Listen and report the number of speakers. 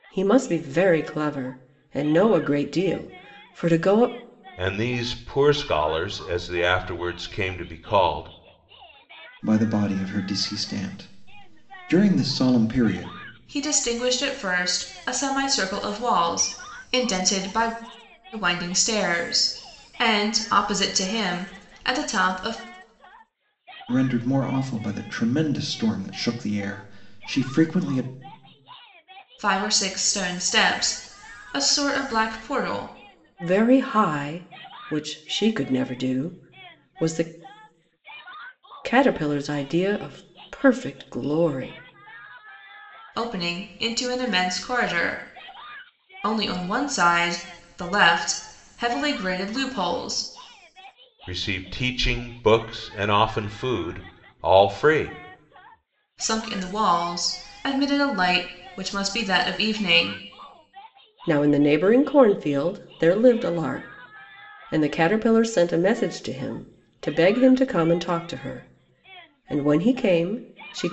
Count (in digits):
4